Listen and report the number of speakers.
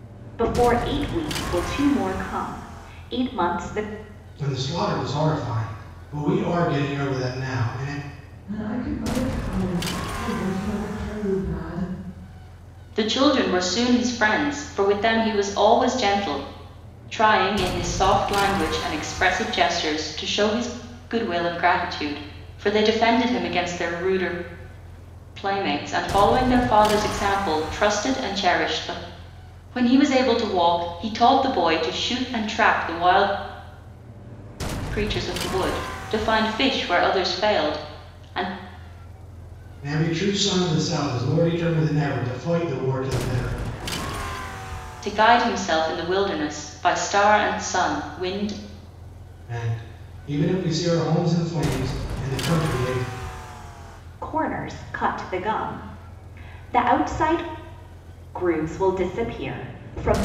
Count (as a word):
four